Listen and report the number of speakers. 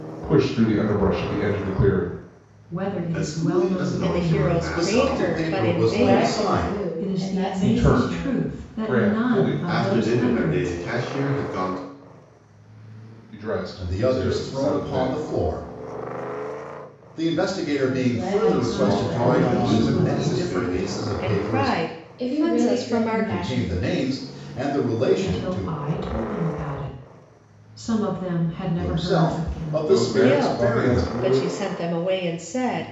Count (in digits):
6